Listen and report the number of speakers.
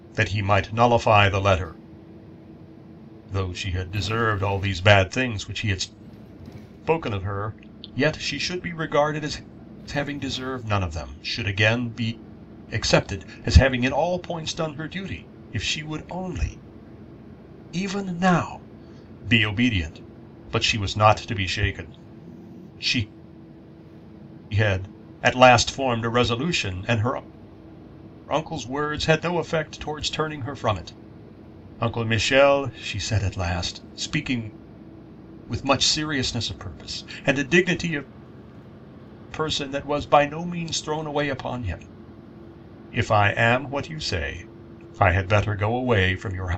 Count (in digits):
1